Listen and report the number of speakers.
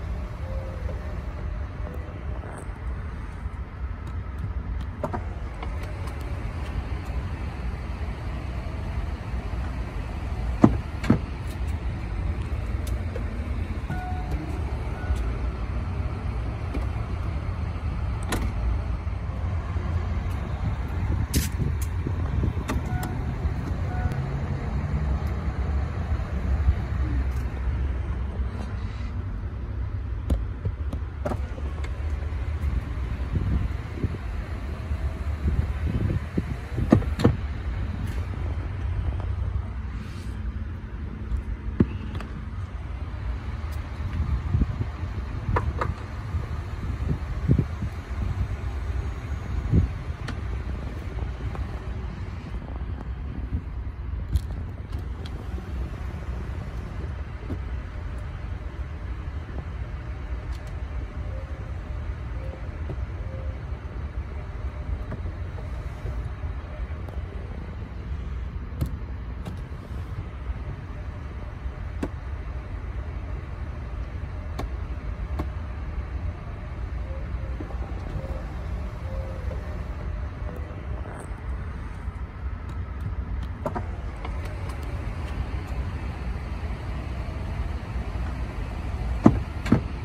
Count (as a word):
zero